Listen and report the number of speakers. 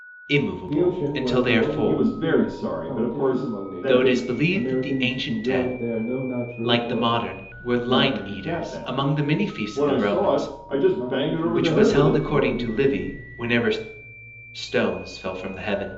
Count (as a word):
three